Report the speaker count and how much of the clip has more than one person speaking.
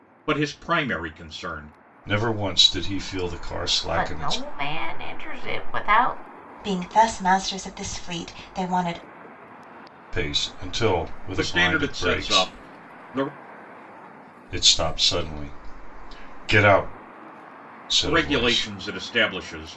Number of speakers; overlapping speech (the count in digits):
4, about 12%